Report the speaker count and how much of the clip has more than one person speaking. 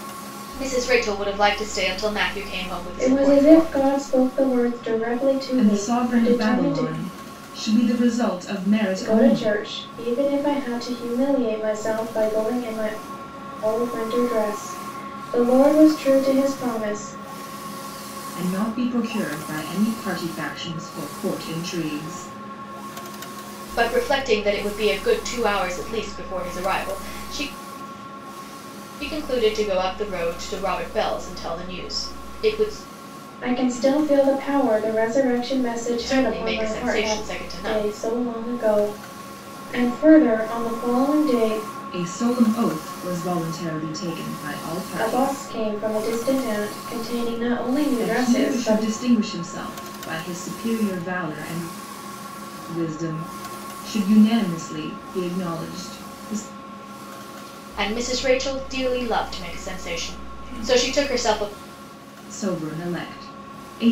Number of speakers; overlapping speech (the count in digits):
3, about 9%